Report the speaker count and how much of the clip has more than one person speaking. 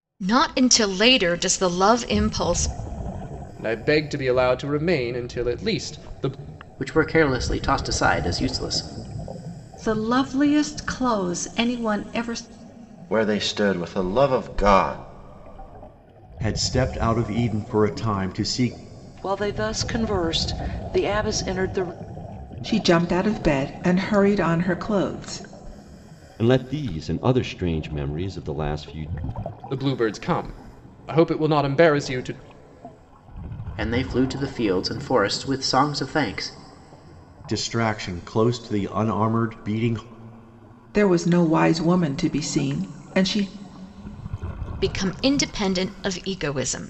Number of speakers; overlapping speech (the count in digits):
9, no overlap